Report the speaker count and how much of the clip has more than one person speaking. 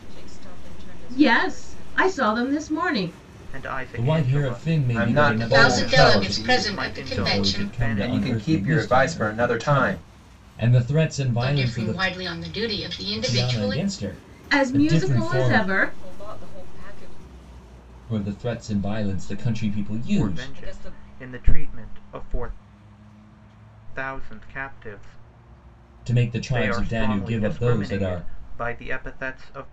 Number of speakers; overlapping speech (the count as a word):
six, about 47%